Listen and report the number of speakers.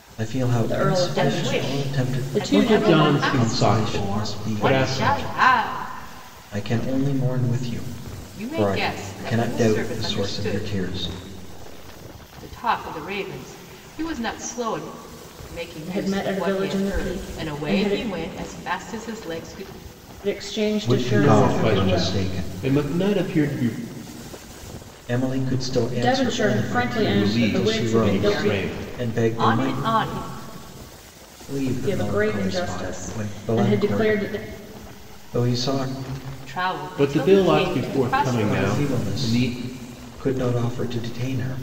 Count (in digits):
4